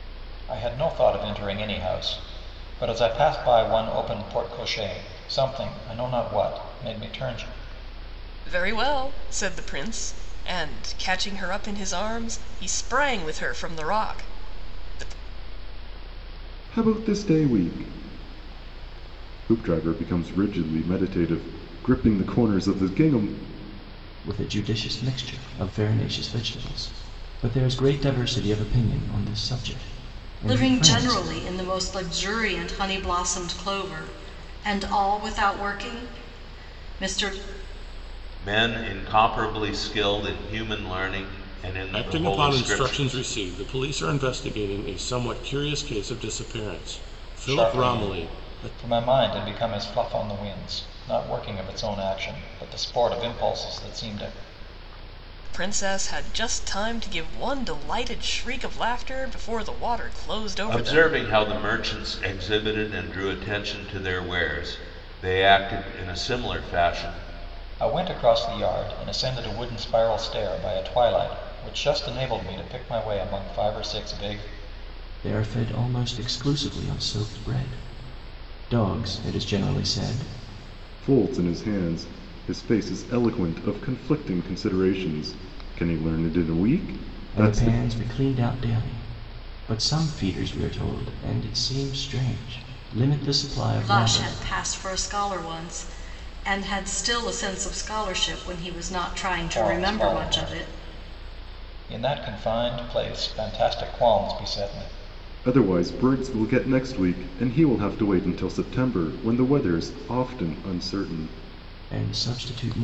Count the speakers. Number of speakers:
7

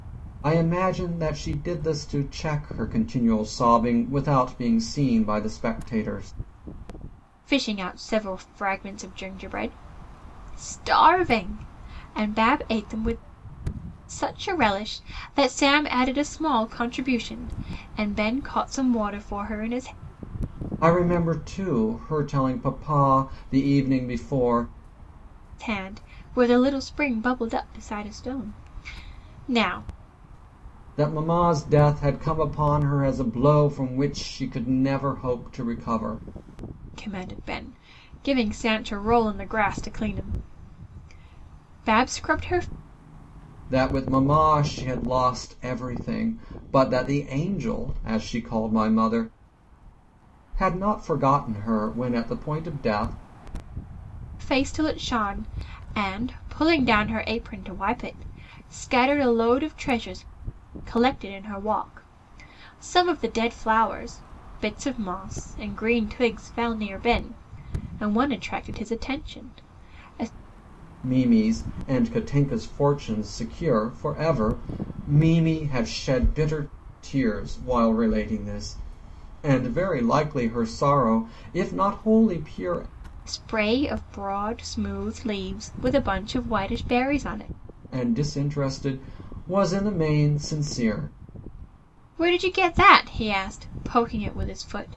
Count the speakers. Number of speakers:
2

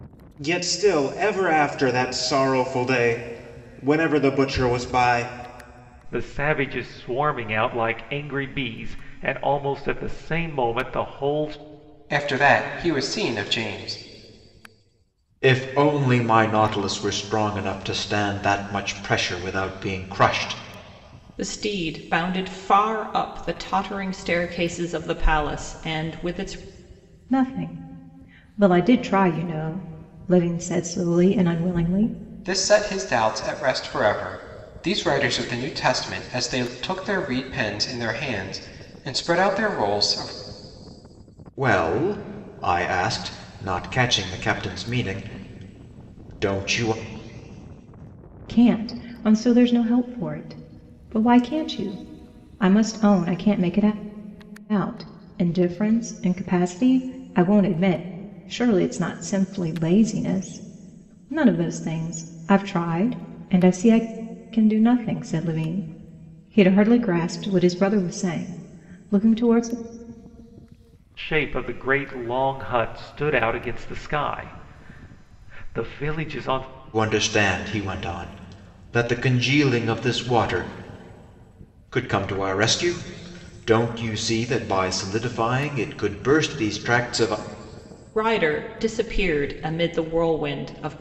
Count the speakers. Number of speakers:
6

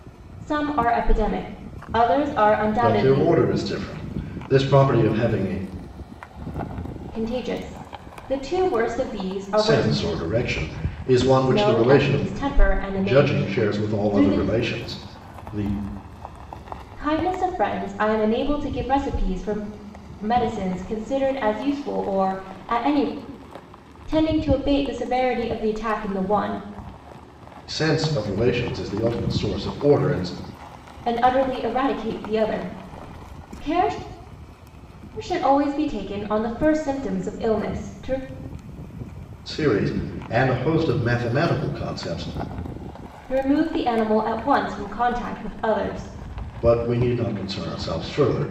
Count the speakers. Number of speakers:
2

